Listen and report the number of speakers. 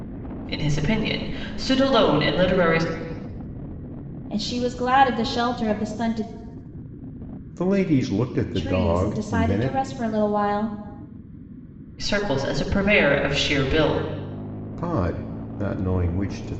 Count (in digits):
3